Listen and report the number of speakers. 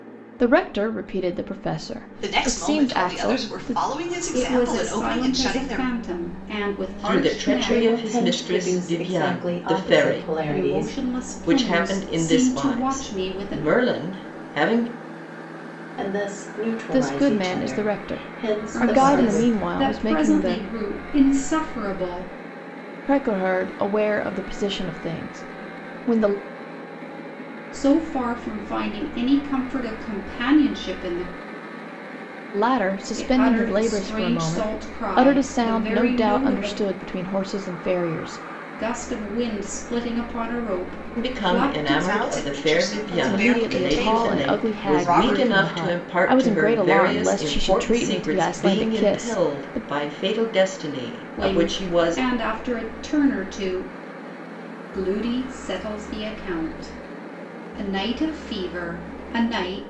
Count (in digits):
5